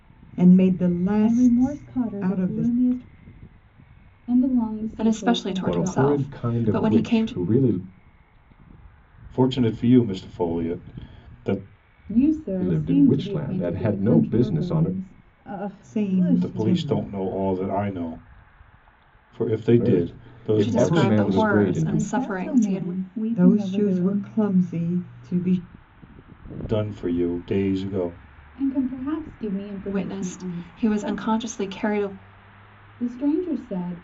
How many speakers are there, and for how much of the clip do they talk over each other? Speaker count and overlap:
six, about 41%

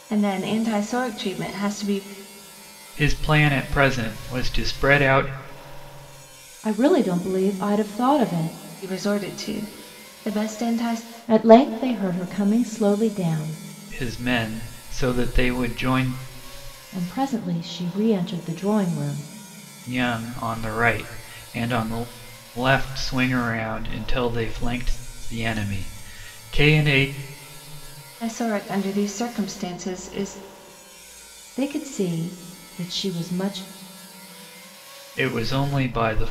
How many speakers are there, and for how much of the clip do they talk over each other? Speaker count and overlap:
three, no overlap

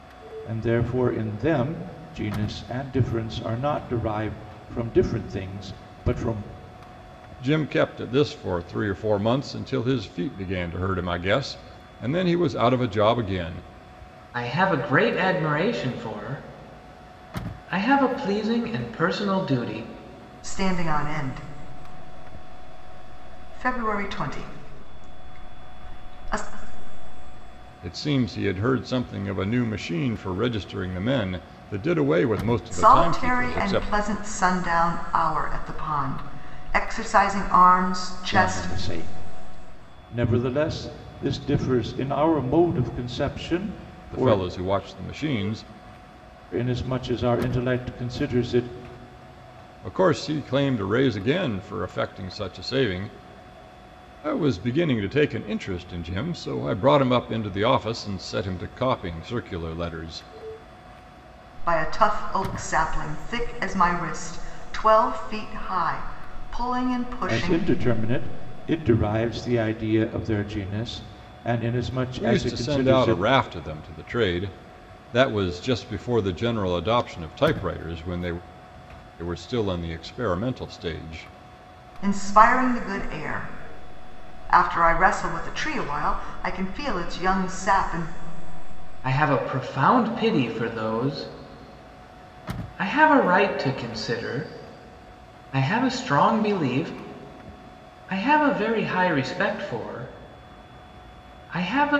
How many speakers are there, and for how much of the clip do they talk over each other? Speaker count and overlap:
four, about 4%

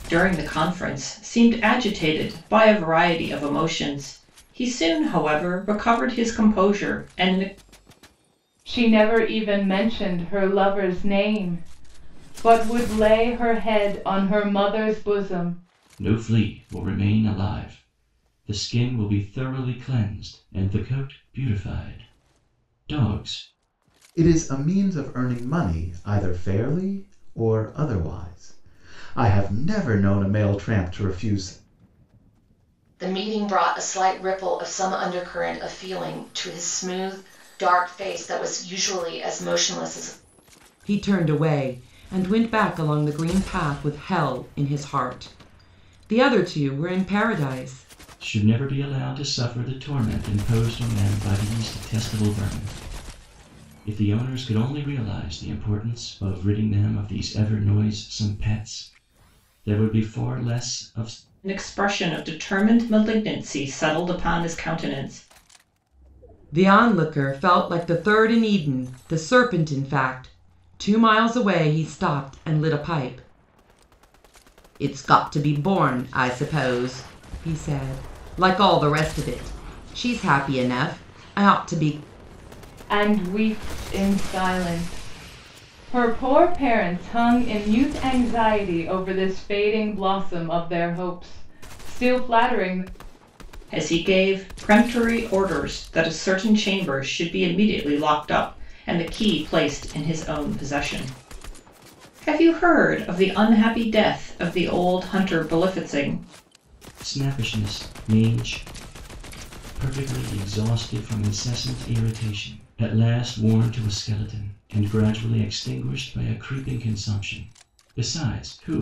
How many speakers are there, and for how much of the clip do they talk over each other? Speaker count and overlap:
six, no overlap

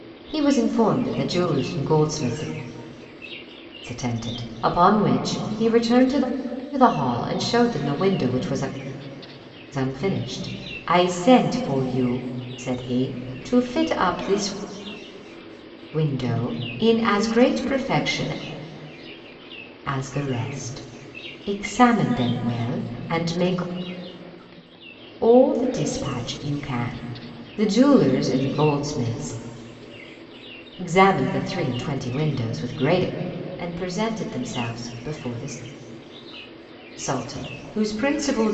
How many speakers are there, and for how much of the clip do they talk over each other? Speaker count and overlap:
one, no overlap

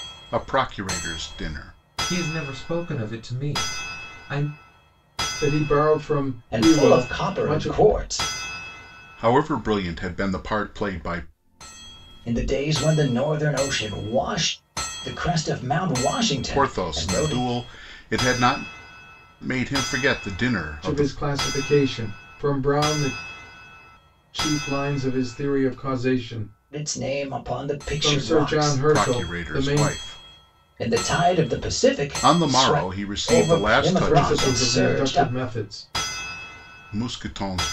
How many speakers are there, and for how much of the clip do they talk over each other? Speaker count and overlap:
four, about 20%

